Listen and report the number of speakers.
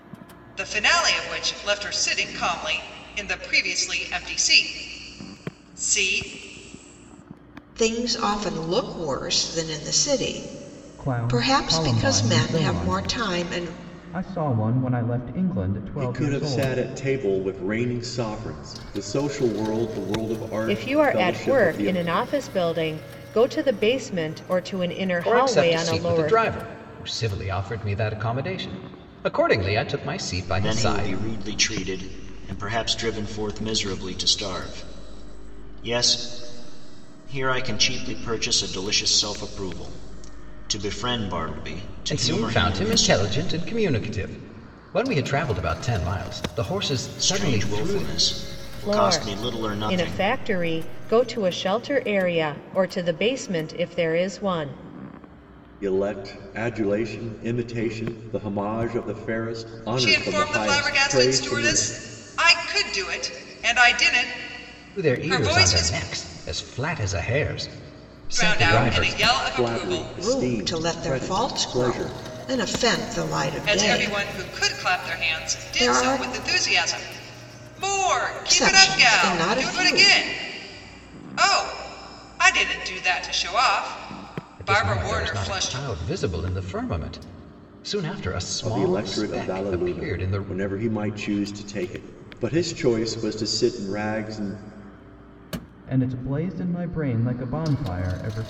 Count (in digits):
7